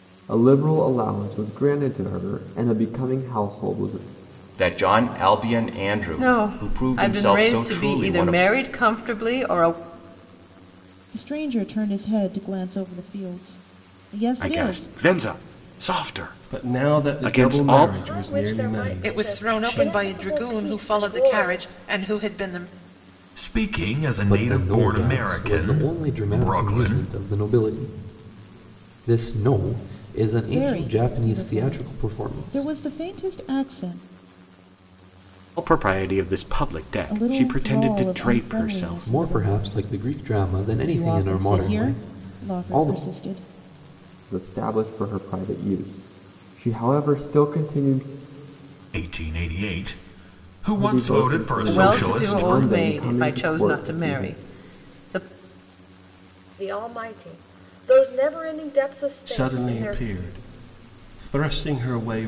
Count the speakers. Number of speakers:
10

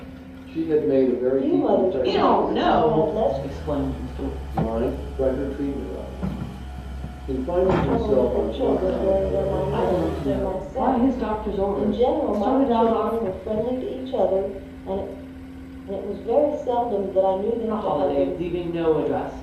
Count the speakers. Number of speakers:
3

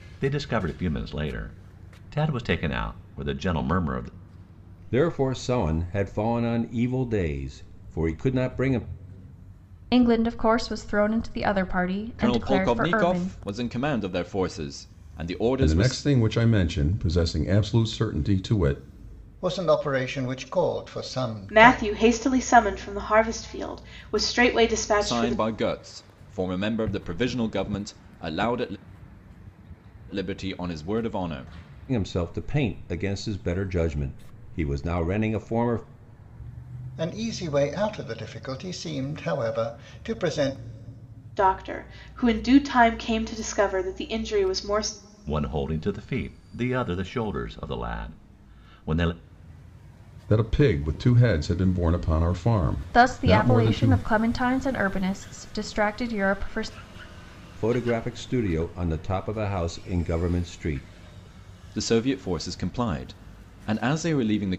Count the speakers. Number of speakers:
7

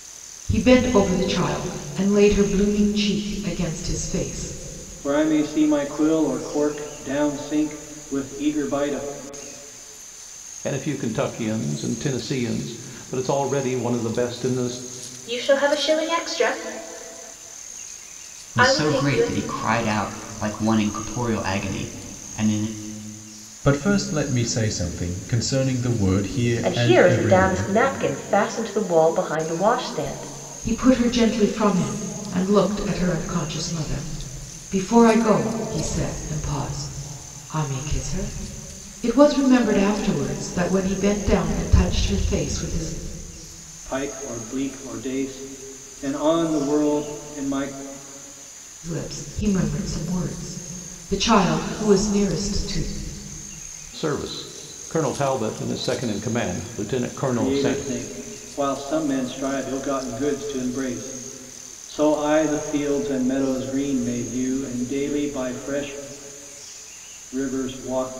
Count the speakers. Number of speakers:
7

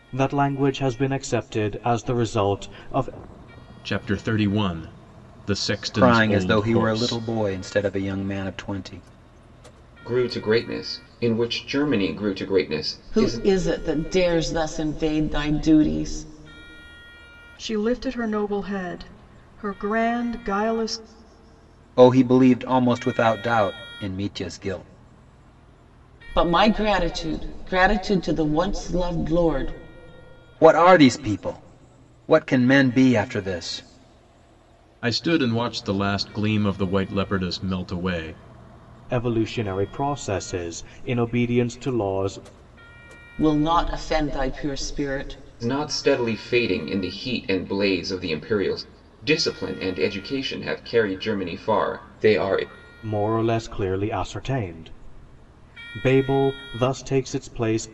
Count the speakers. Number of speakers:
6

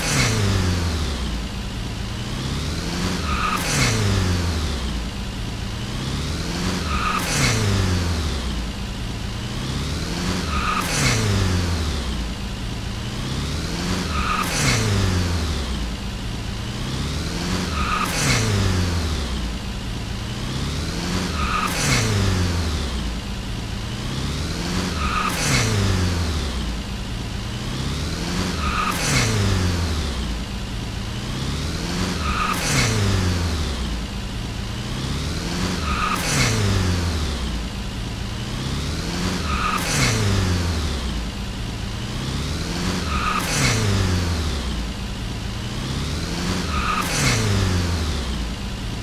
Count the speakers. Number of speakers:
0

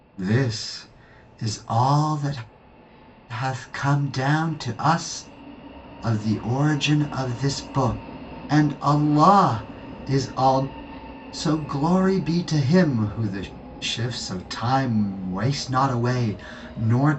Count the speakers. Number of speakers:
1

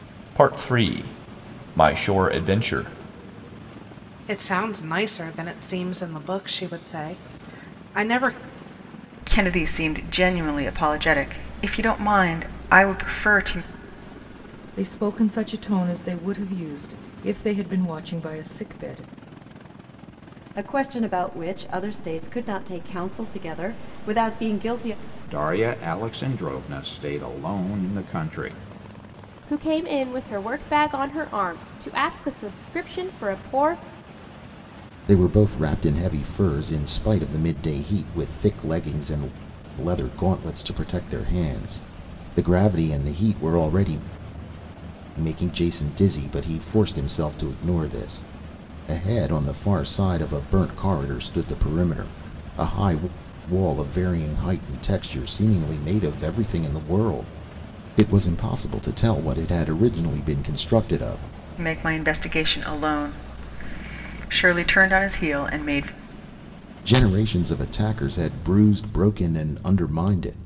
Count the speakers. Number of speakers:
8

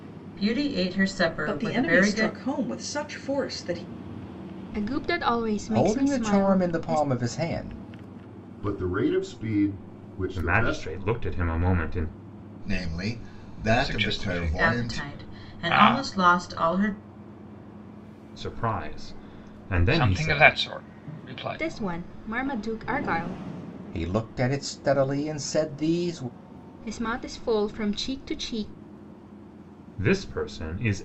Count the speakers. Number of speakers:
8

